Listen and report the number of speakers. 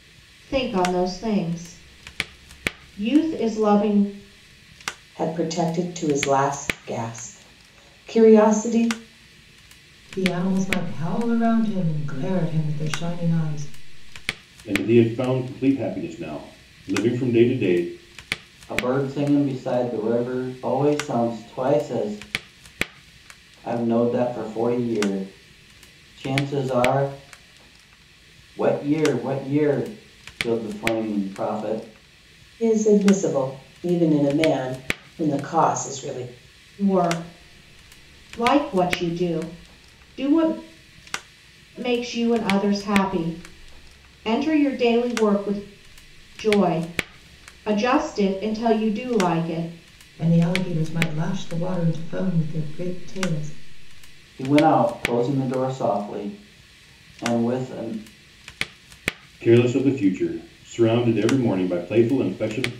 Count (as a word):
five